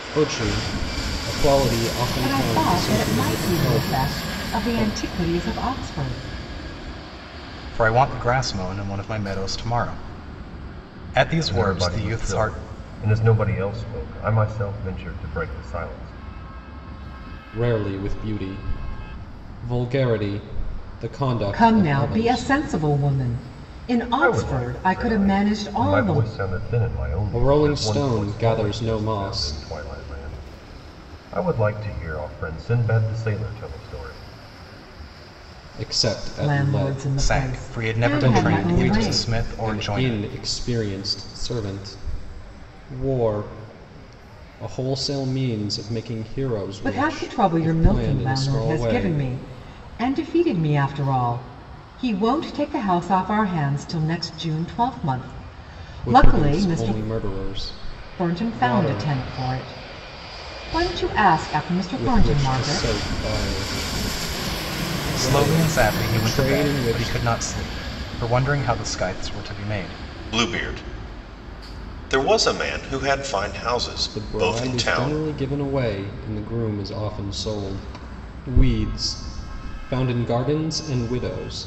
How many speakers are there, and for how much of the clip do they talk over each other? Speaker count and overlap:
four, about 27%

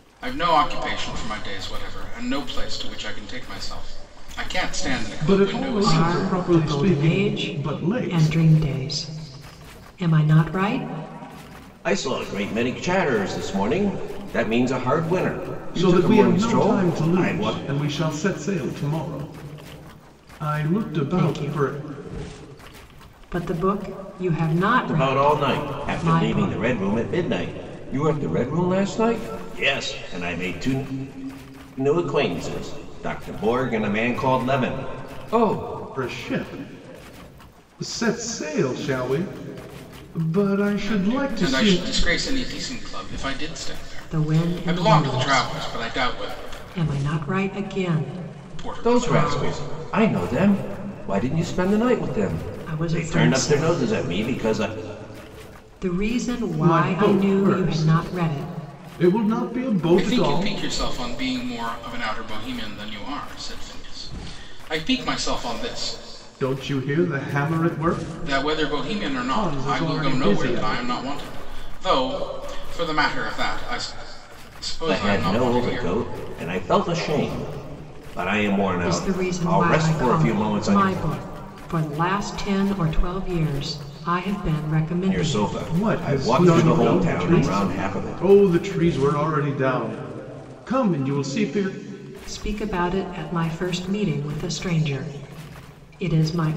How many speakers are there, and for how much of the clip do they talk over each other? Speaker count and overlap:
four, about 27%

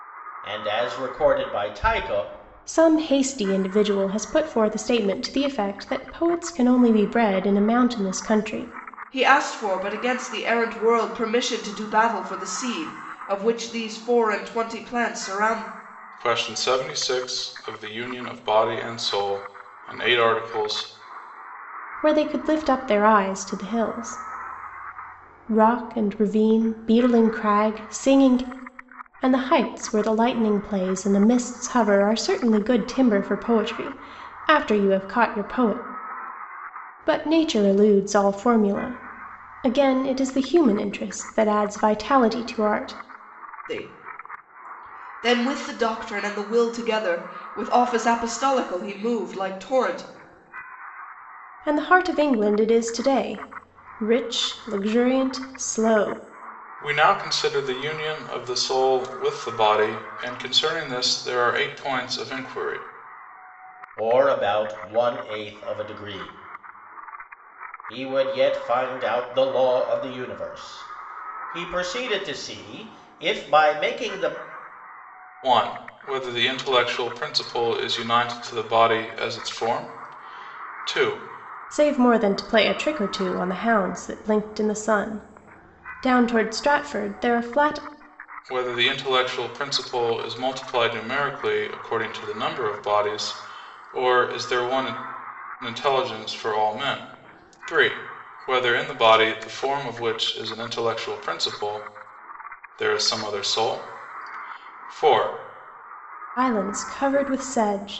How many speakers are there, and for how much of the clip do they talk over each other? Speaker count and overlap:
four, no overlap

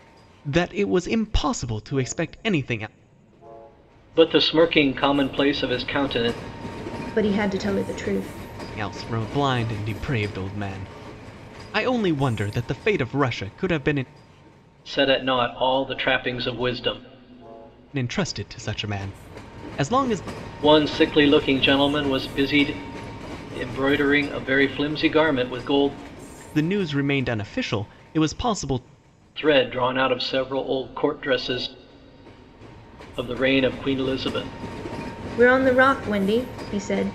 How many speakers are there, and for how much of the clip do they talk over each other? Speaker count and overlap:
three, no overlap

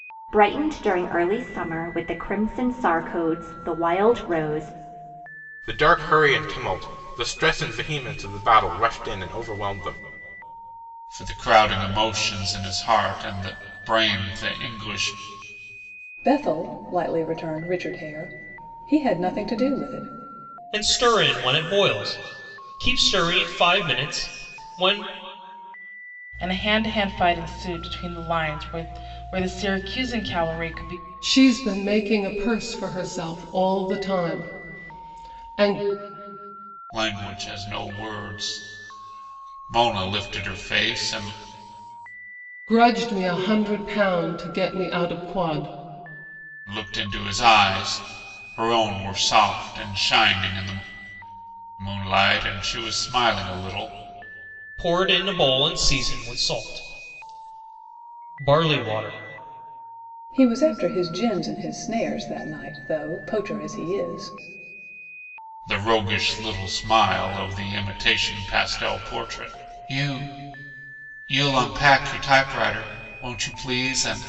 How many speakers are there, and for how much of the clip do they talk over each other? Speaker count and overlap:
seven, no overlap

